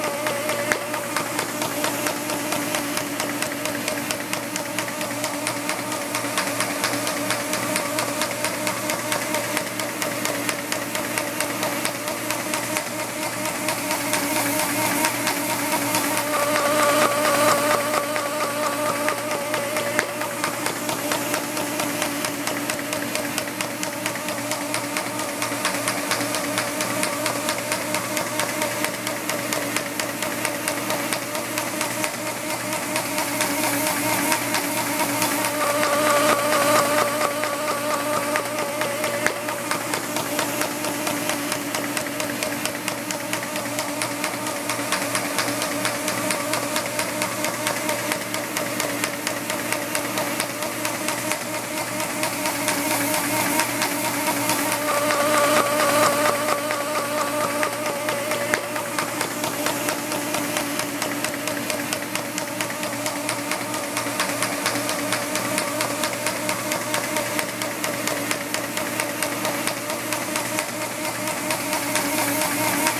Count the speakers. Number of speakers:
0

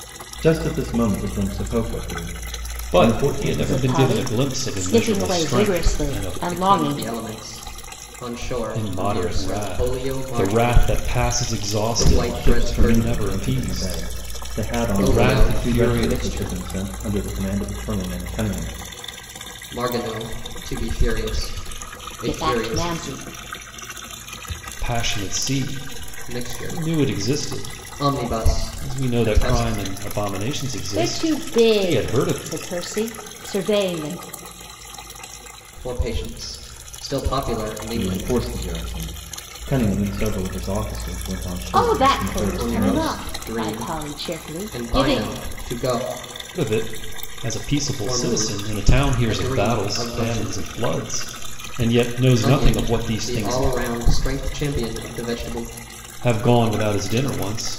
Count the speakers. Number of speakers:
4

